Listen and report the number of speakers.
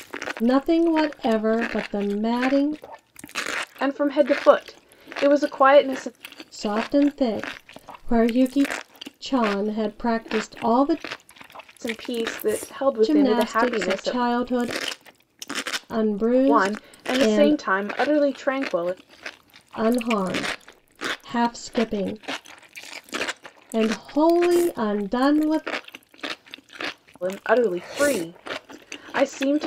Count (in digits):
2